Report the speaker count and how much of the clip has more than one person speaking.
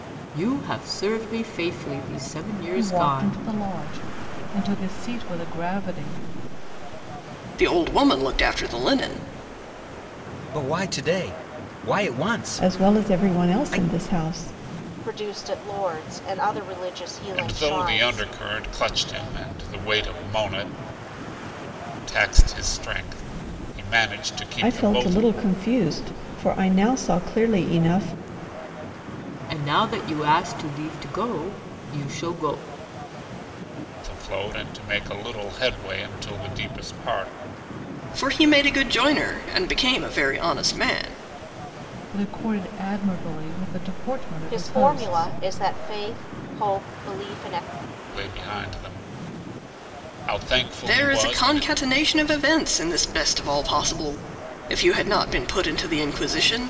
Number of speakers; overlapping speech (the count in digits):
7, about 10%